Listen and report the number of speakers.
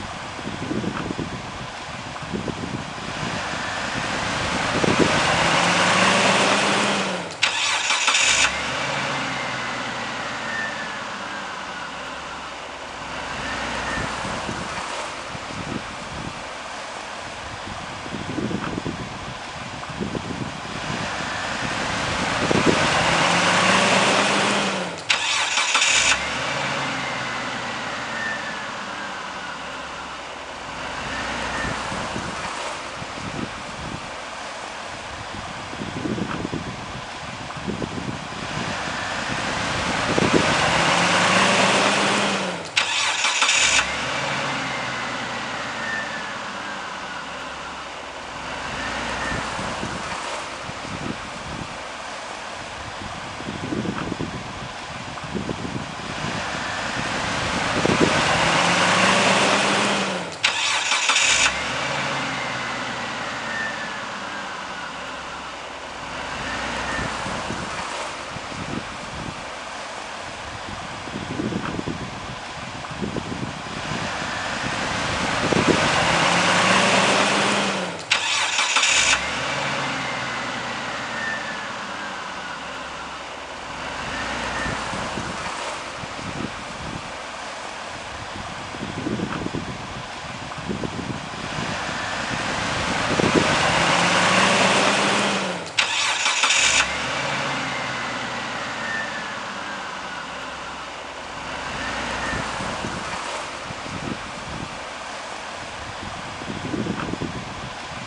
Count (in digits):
0